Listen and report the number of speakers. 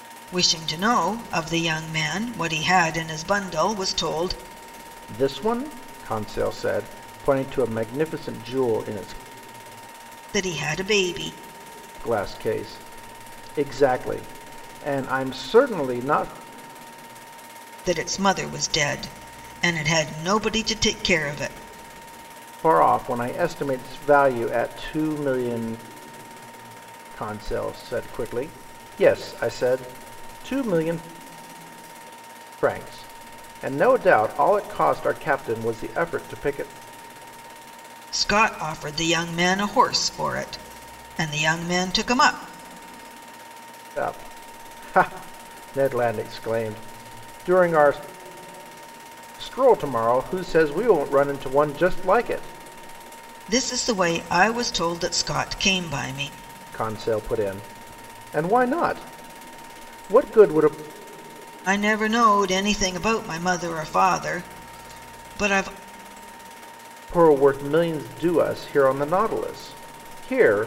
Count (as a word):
two